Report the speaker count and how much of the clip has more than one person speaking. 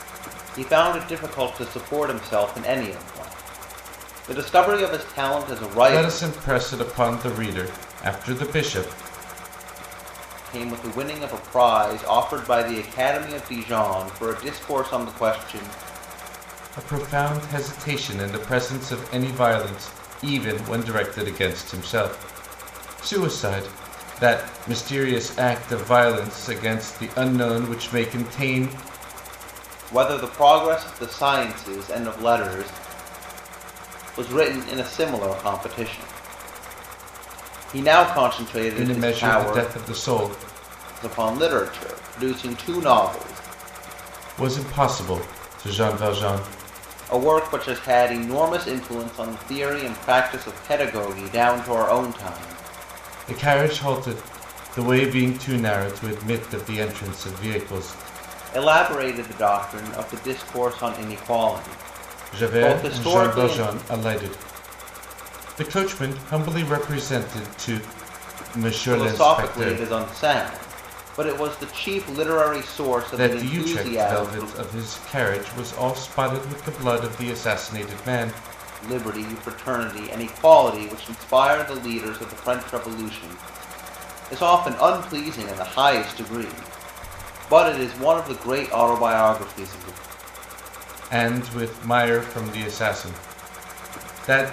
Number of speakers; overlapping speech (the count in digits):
2, about 6%